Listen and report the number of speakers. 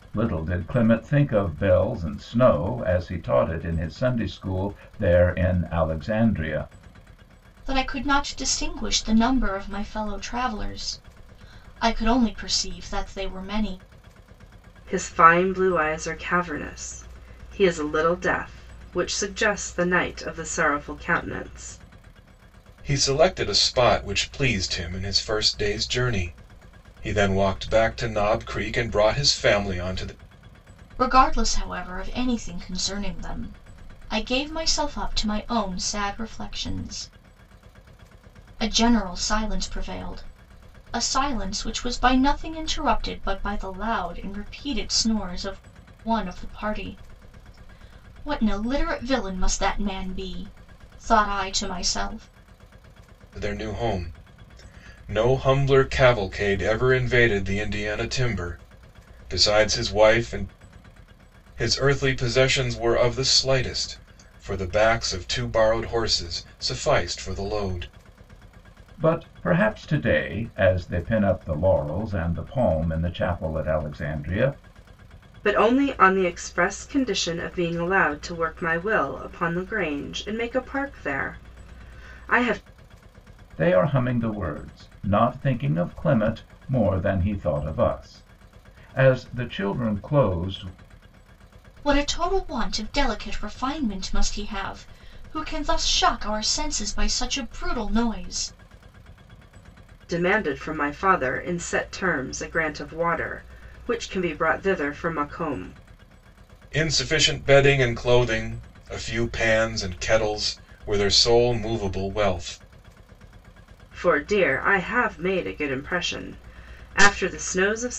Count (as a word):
four